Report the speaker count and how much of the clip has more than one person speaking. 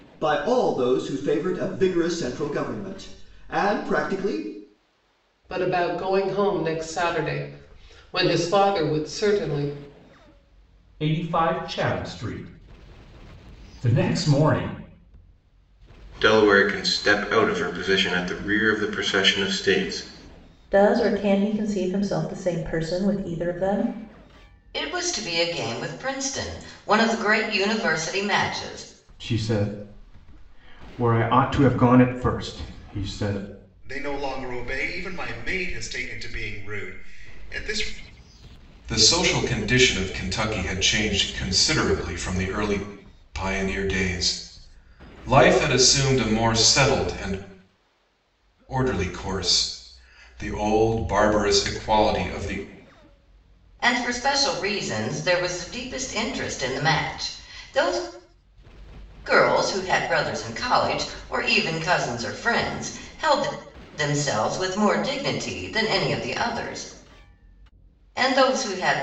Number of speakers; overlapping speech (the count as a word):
nine, no overlap